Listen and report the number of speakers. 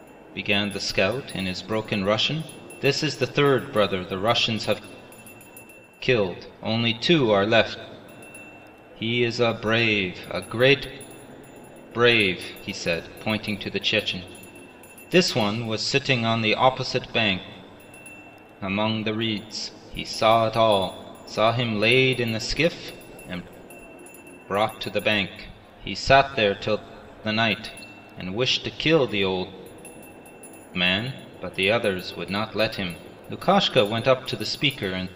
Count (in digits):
1